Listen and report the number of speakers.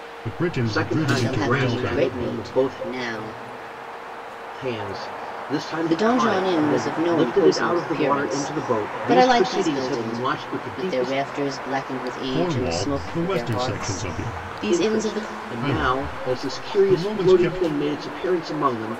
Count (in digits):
3